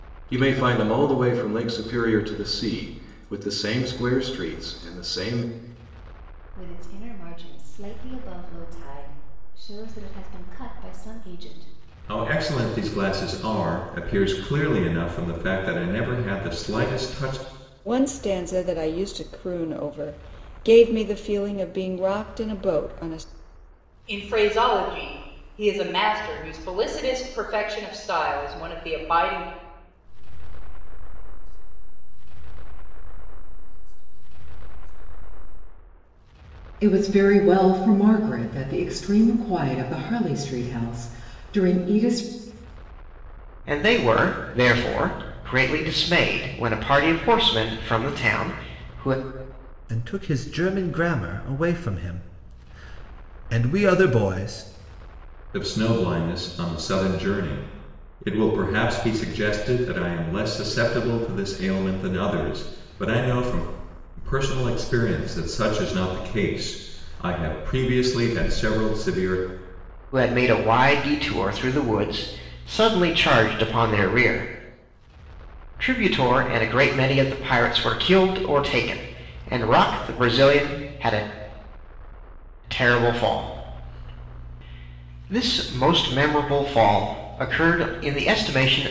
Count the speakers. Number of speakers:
9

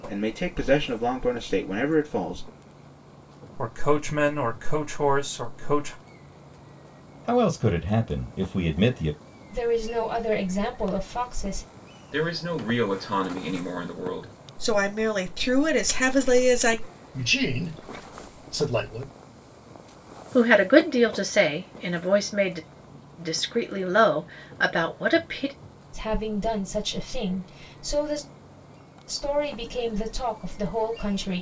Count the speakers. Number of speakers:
8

